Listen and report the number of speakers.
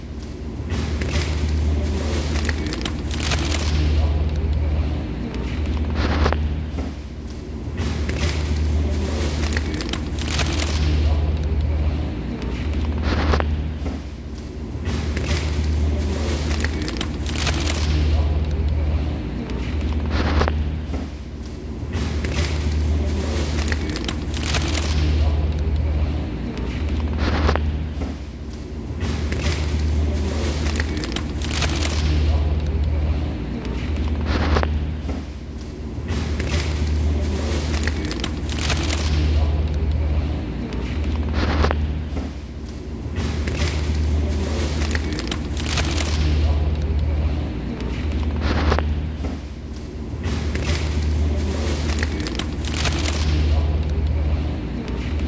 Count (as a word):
zero